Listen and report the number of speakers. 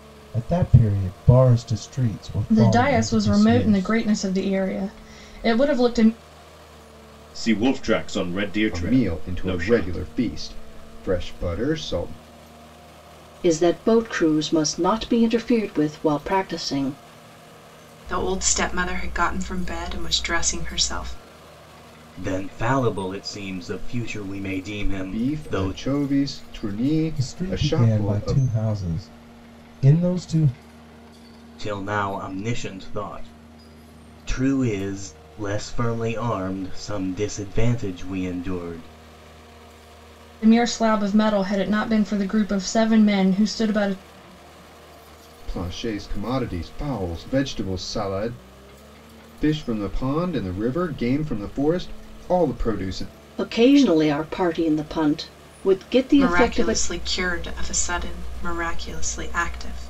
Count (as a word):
seven